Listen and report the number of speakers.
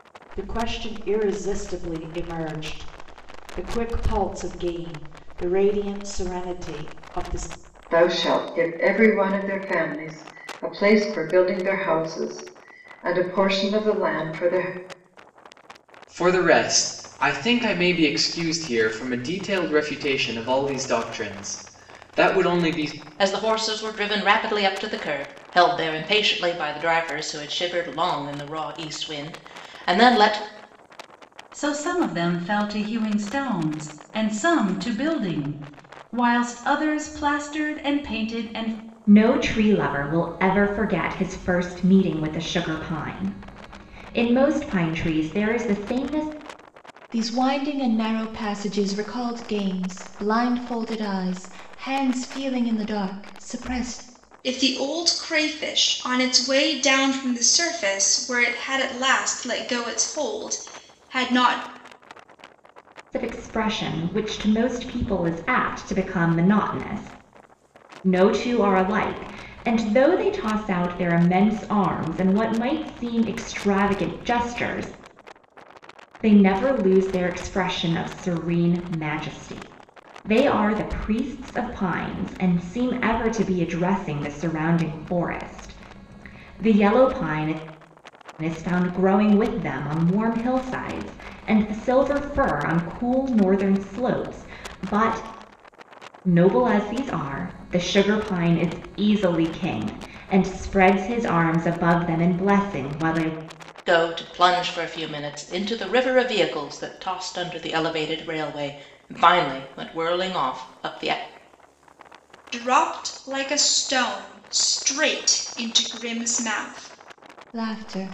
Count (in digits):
8